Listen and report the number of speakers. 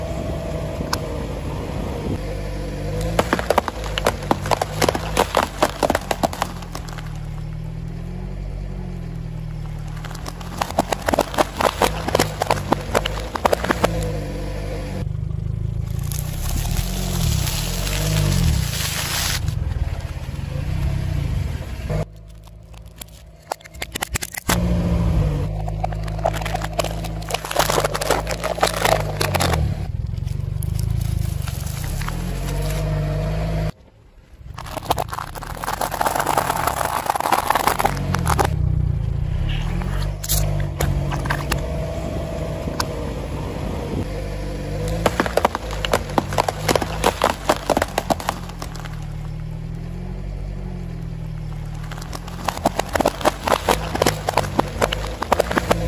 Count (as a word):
zero